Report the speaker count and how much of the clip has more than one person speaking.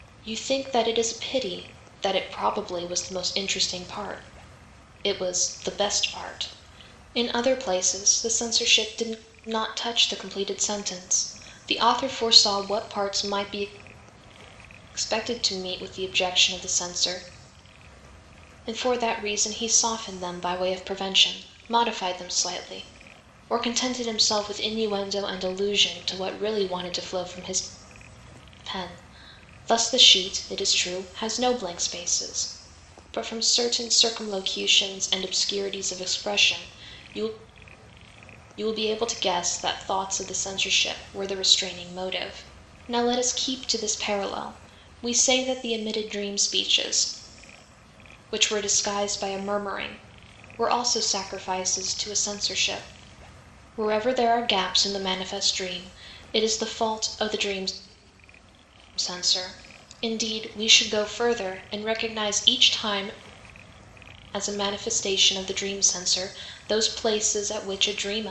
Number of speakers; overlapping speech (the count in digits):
1, no overlap